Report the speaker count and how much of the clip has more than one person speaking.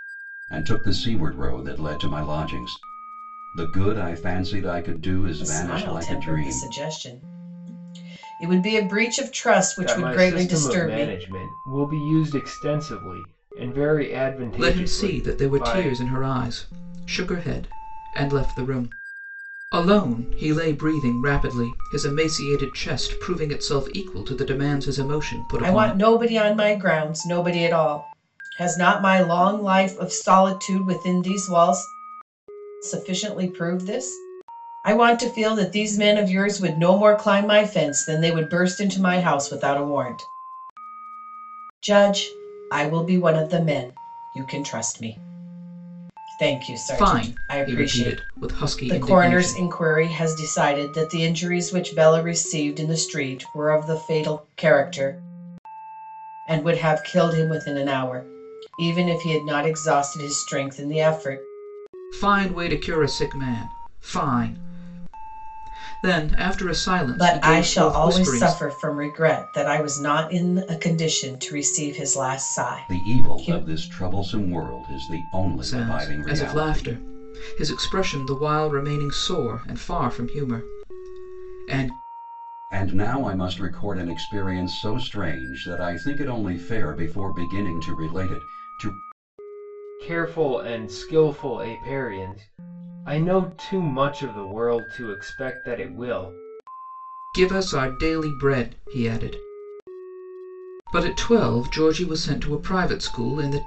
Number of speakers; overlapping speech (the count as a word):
four, about 10%